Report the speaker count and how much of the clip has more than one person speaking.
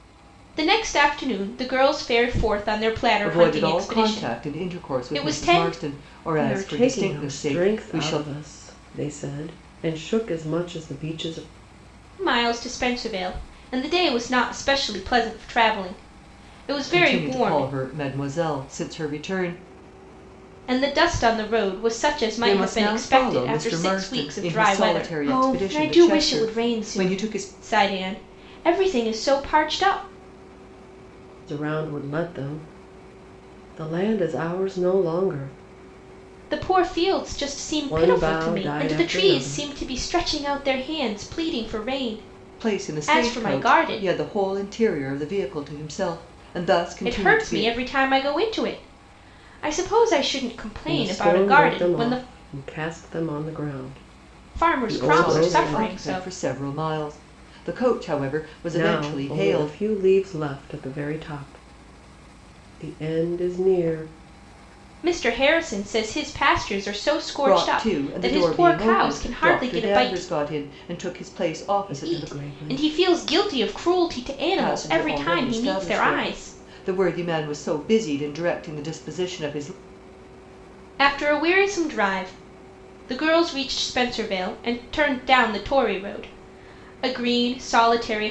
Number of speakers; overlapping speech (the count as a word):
three, about 28%